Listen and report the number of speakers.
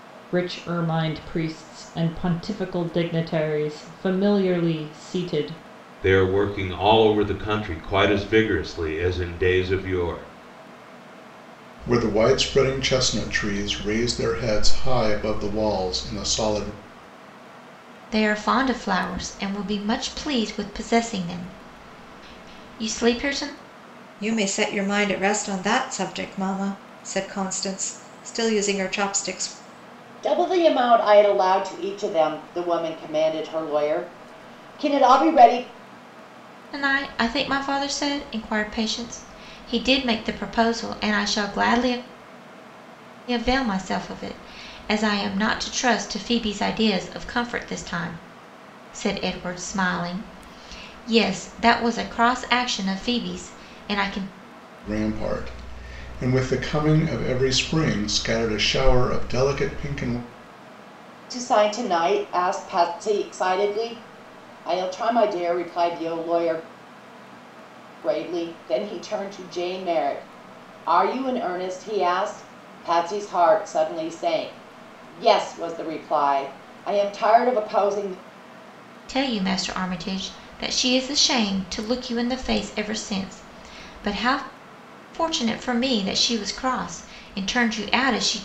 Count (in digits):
6